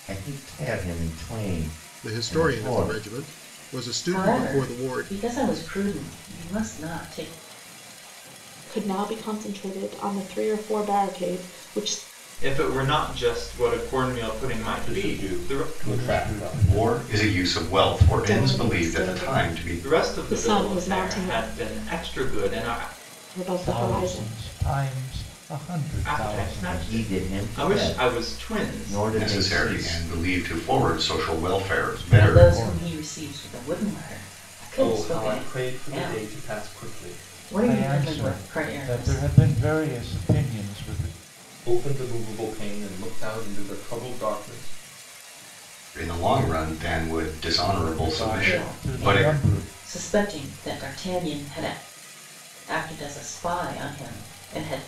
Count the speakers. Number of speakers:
eight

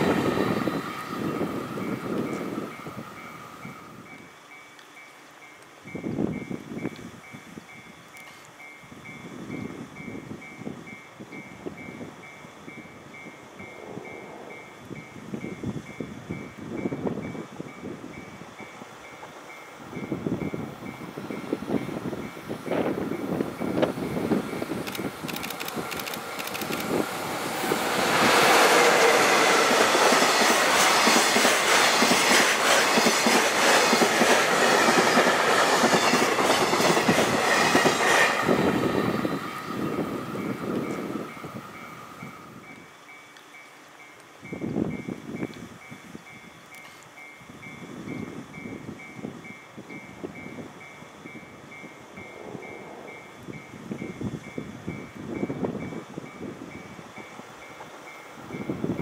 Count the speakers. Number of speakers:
zero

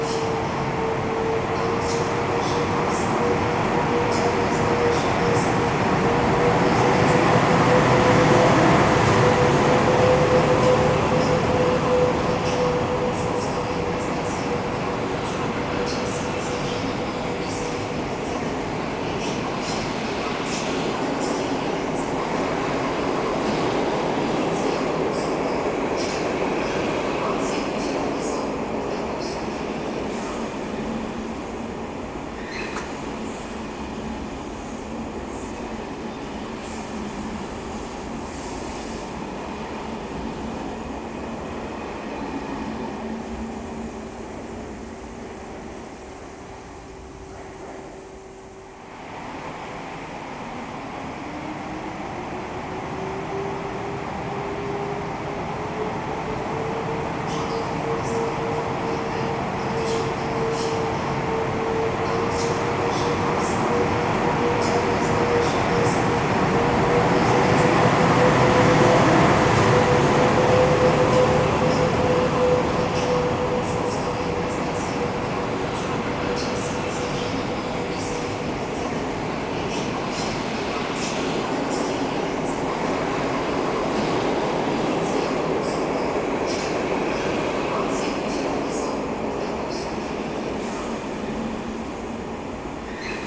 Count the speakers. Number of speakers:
zero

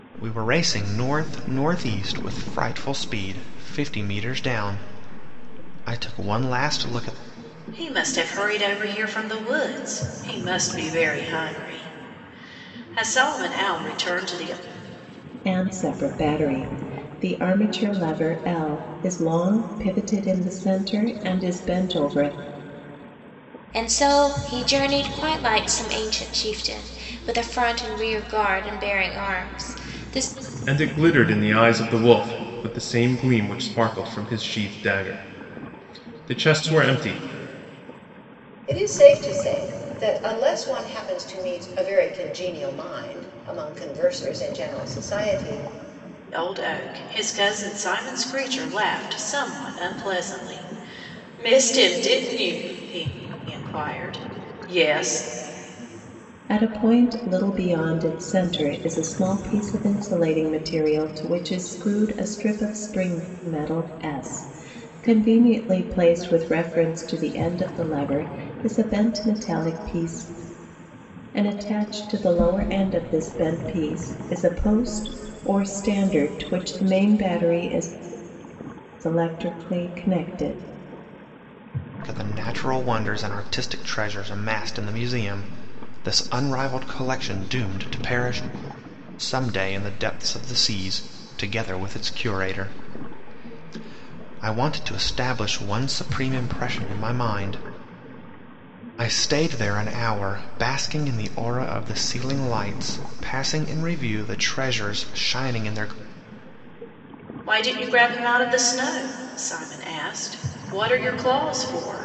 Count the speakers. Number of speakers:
six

